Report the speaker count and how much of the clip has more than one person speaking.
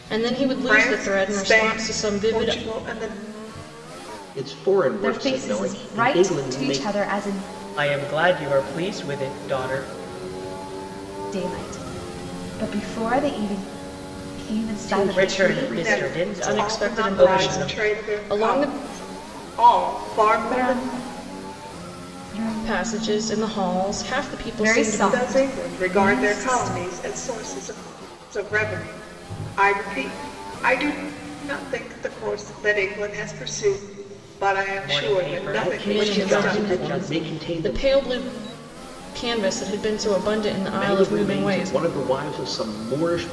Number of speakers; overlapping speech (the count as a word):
five, about 38%